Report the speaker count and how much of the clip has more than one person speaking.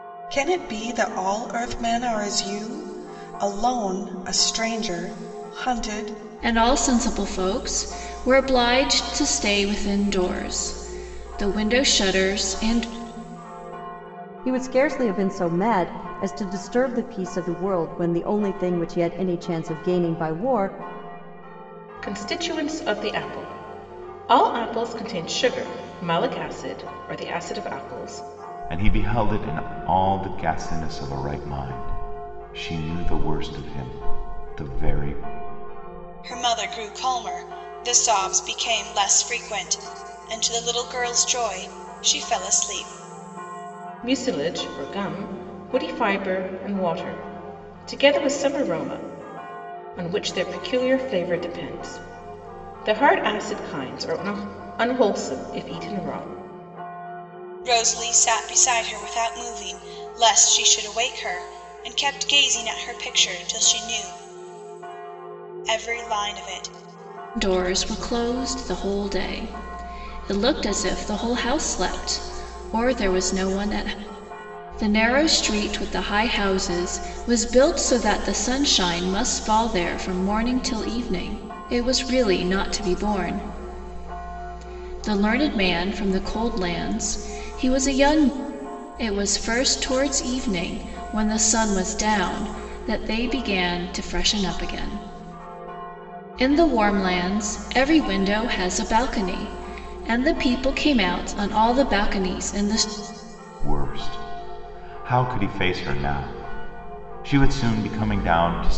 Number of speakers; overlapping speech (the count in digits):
6, no overlap